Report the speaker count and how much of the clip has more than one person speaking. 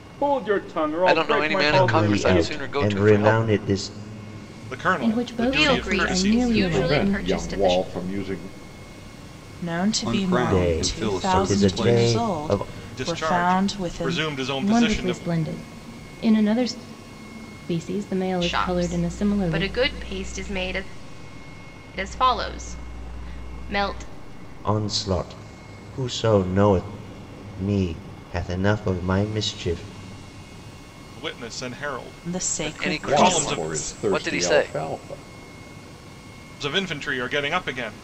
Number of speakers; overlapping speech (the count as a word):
nine, about 36%